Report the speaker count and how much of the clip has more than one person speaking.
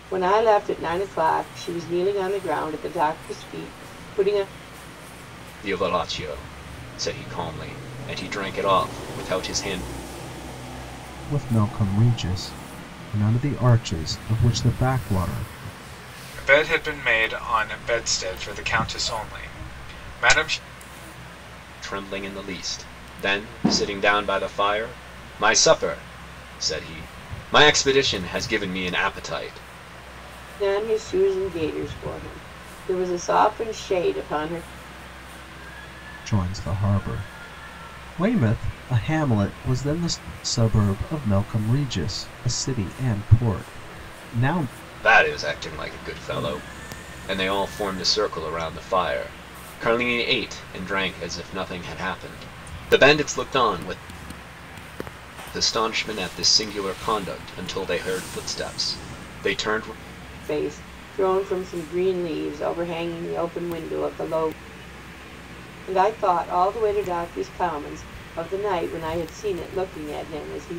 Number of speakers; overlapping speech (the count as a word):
four, no overlap